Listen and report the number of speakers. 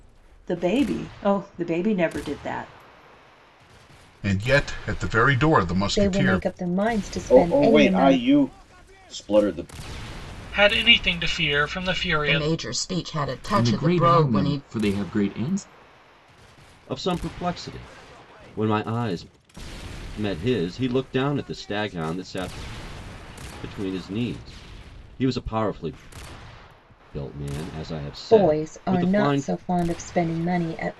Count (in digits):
8